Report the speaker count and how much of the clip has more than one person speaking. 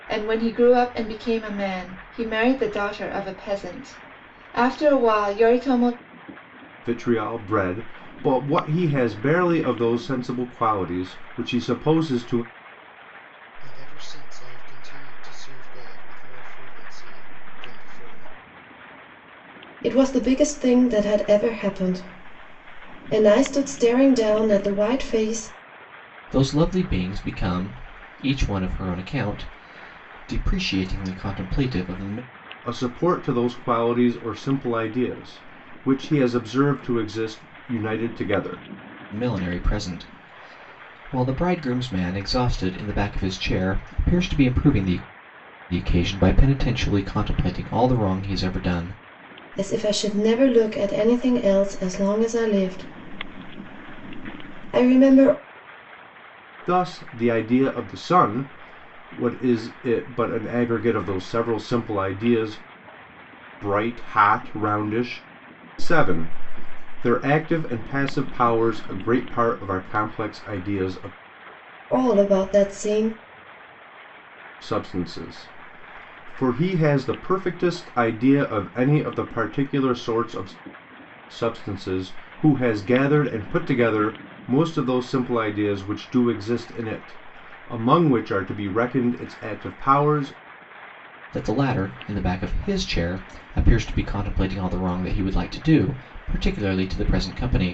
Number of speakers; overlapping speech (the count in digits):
5, no overlap